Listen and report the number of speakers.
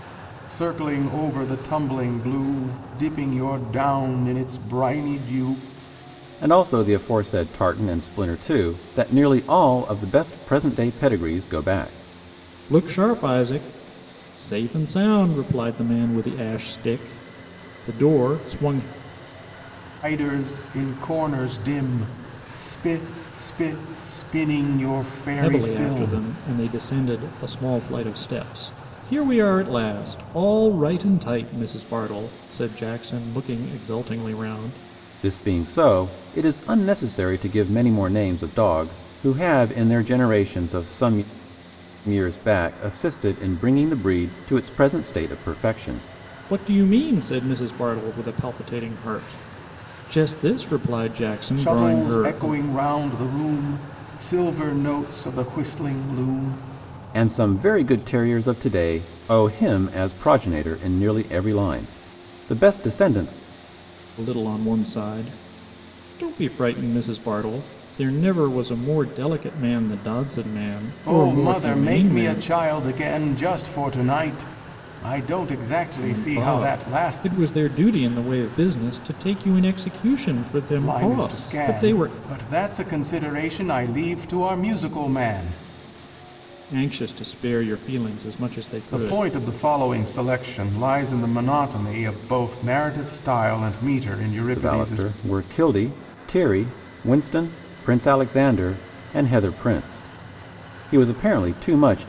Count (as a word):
three